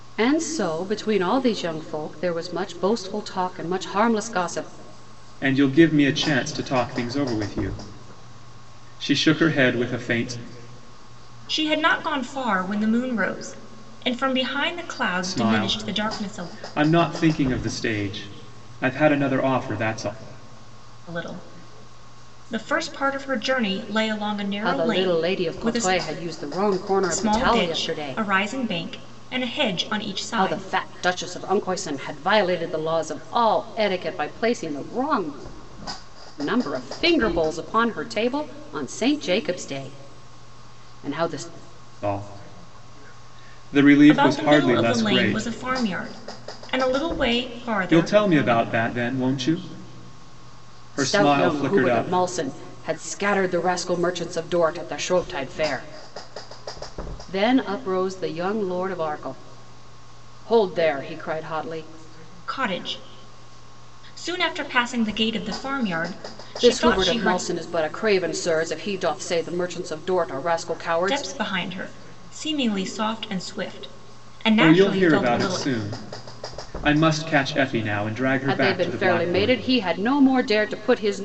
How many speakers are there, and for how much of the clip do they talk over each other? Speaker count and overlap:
3, about 14%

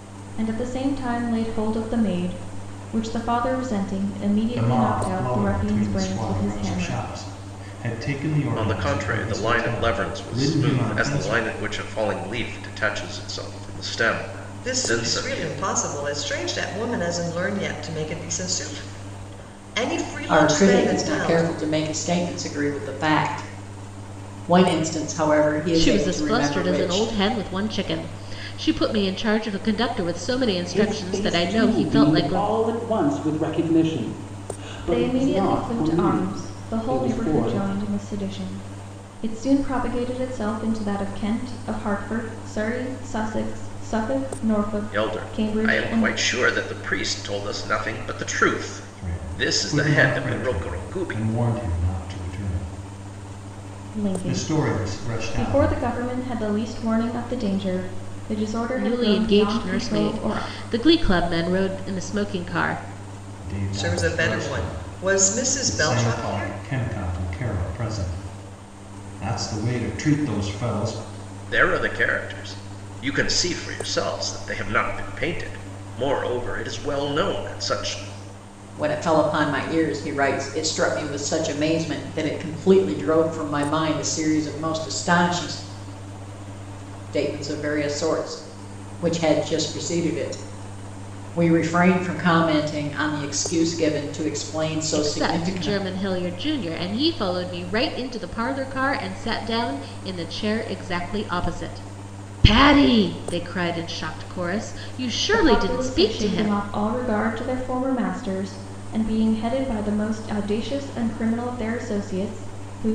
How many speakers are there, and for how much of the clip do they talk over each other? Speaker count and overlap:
7, about 22%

